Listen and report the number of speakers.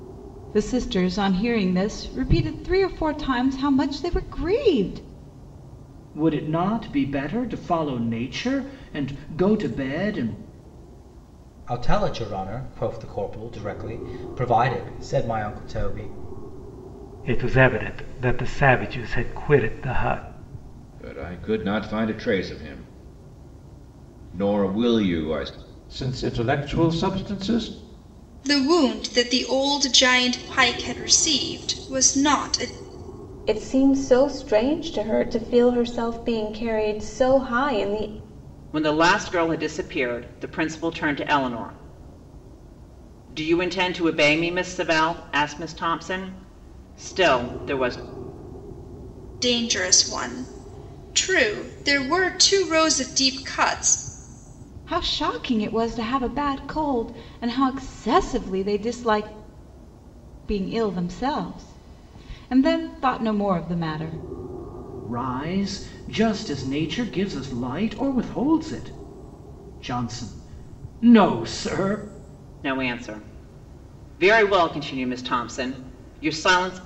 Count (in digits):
9